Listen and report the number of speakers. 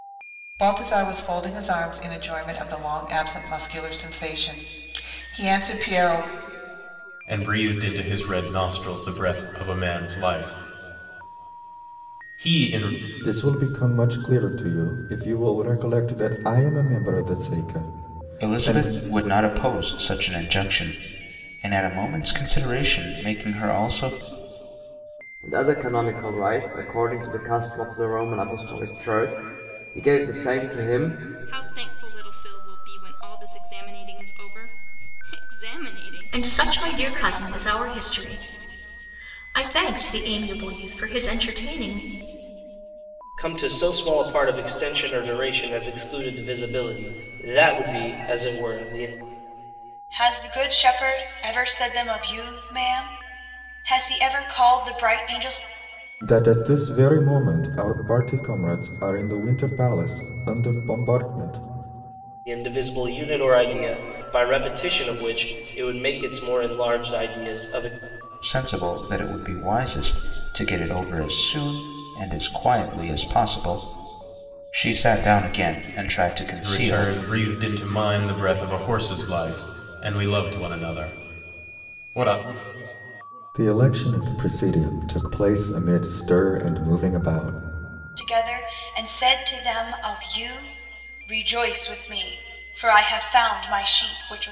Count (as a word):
nine